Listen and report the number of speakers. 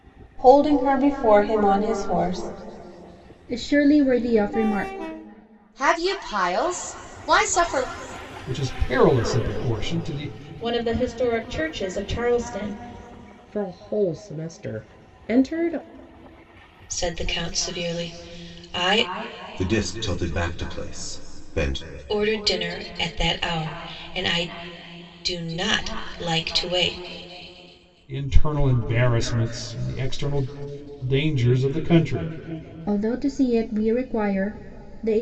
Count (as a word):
eight